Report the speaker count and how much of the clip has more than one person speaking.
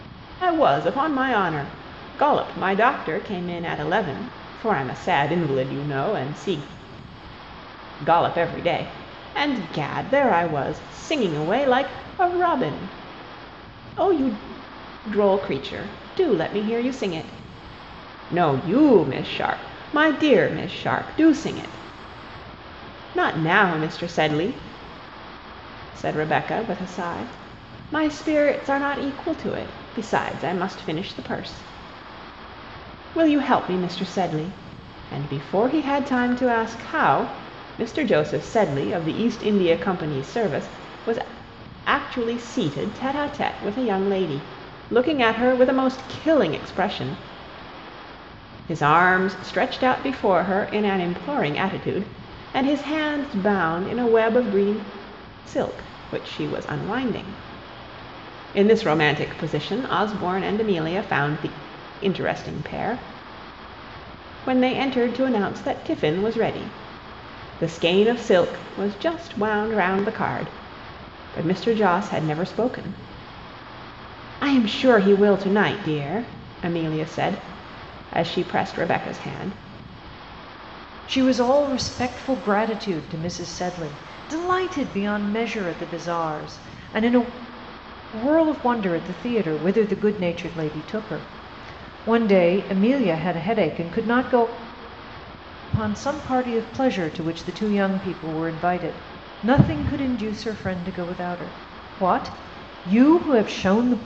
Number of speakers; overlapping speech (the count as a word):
one, no overlap